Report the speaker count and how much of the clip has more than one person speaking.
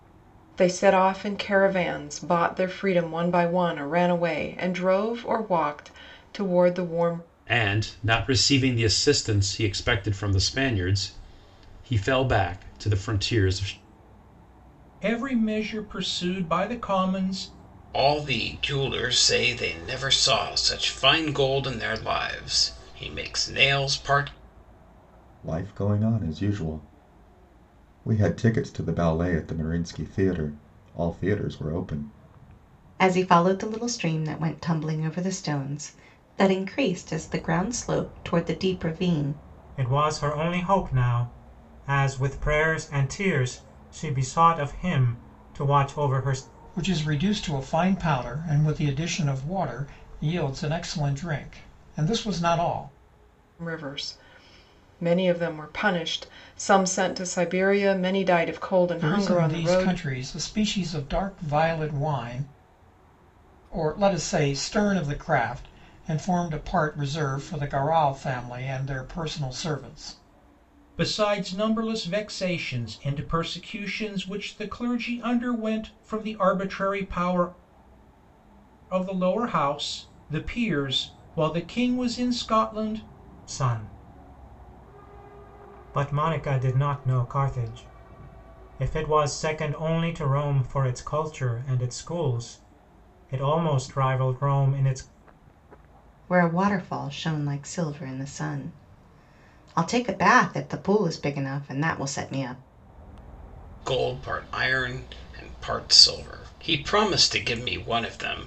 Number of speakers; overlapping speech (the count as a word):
eight, about 1%